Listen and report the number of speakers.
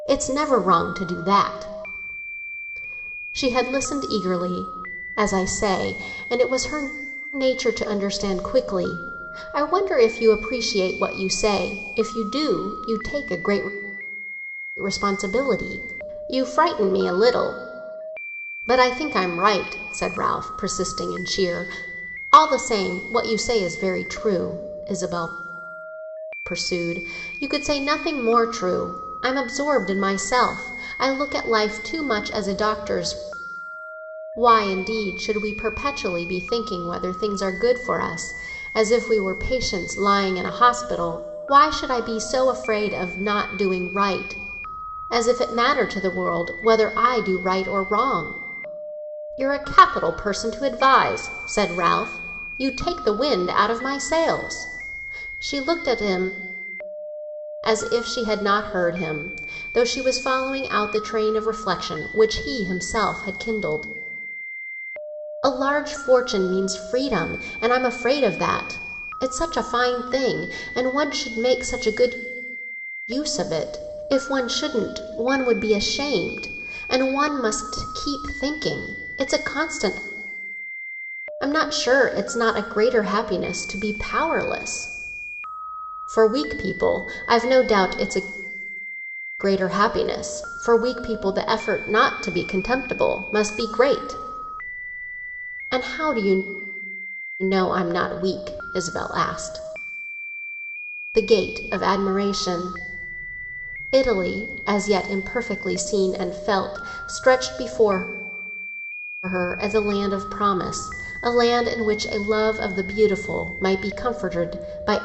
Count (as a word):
one